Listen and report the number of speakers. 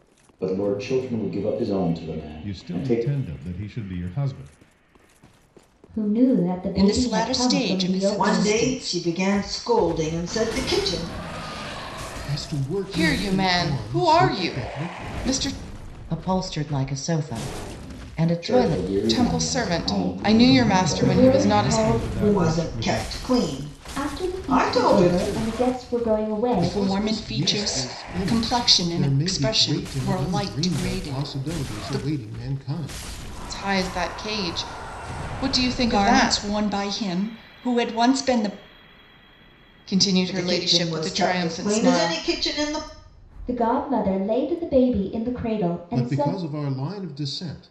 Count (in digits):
8